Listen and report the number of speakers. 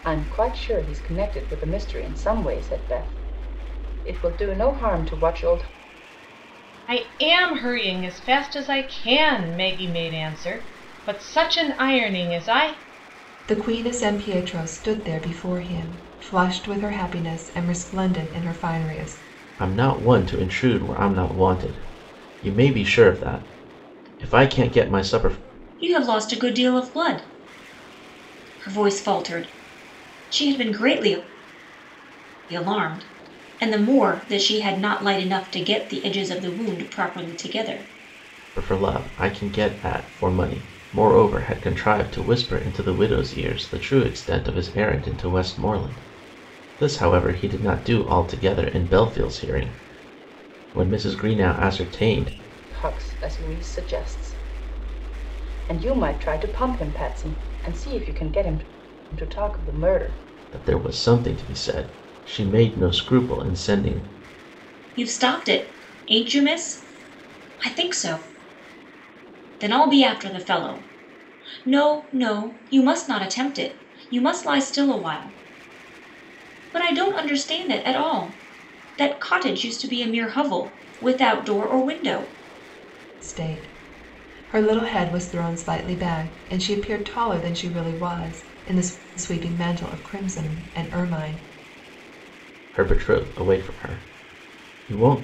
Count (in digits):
5